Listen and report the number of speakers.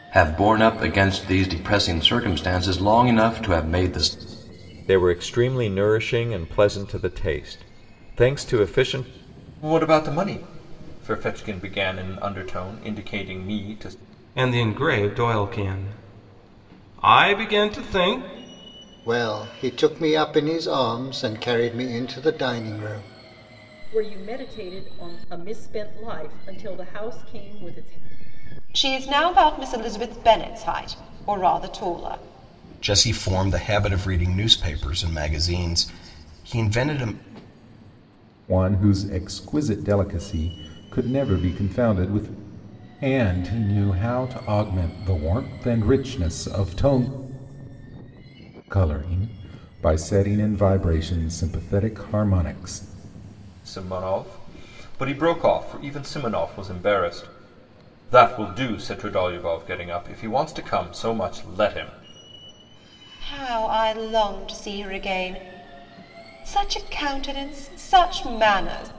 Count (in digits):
9